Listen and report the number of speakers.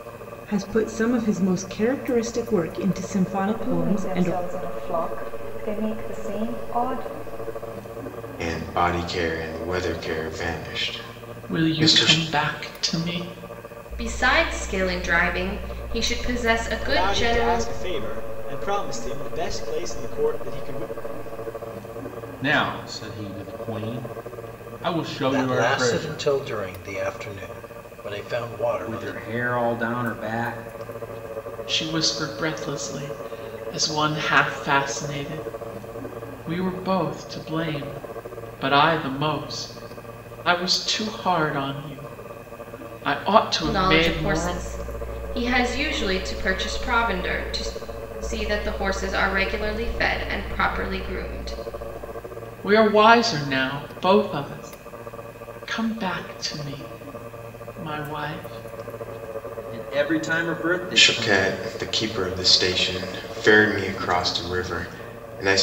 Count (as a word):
nine